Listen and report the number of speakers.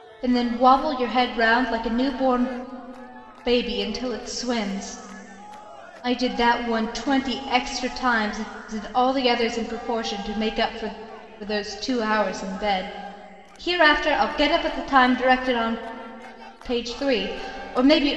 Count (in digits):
1